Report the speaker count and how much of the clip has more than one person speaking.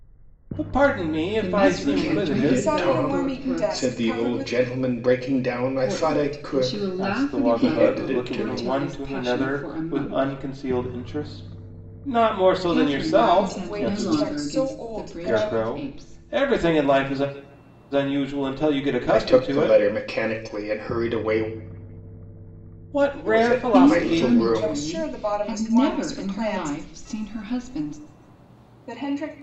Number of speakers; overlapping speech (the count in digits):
4, about 54%